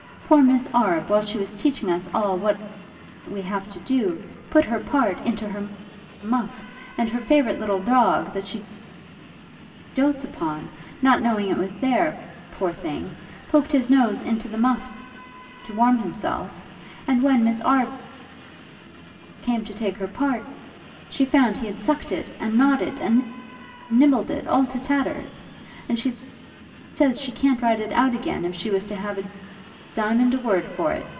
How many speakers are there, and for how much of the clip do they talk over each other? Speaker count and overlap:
one, no overlap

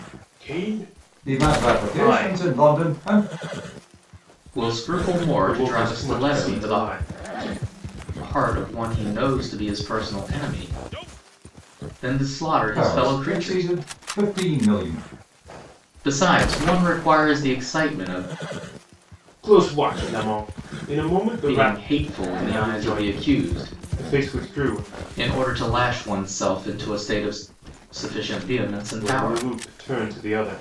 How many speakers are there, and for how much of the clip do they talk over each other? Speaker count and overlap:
three, about 20%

